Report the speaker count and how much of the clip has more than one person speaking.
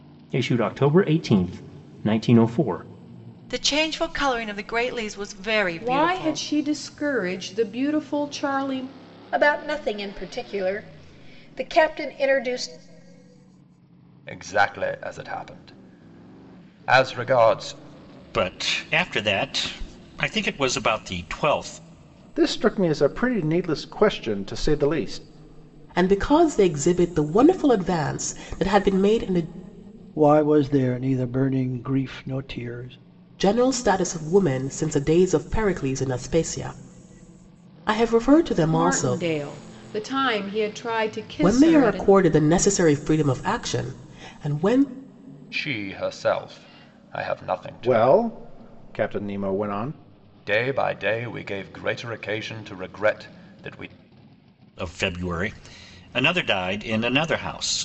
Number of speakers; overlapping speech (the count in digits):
9, about 4%